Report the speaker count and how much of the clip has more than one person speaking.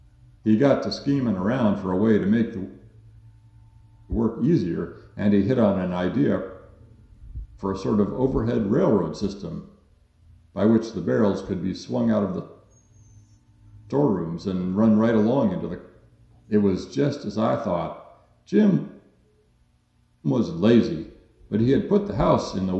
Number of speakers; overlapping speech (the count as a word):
one, no overlap